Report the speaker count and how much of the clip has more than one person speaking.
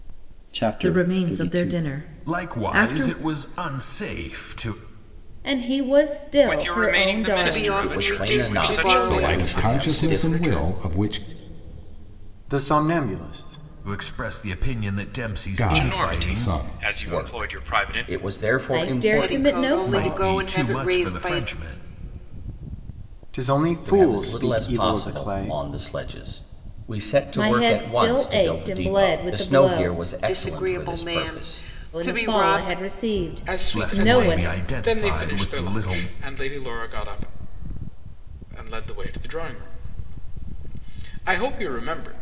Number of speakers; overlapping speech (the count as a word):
ten, about 49%